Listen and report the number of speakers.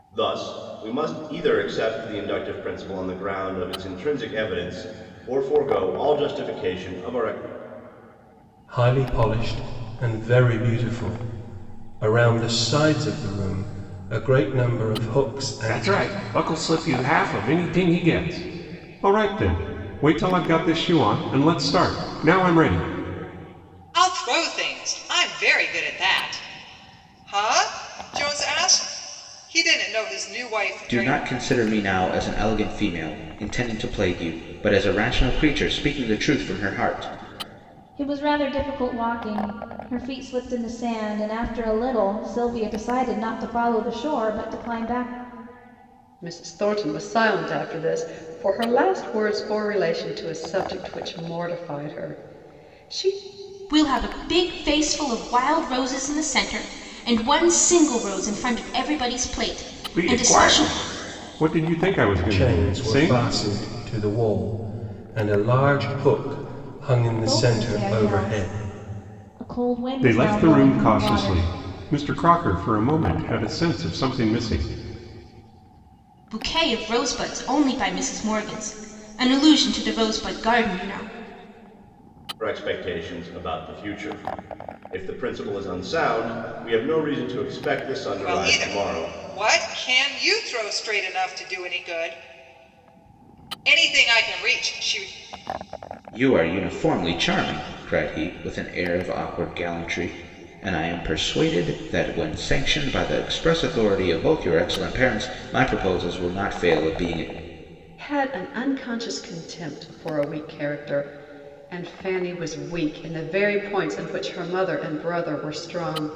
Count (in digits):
8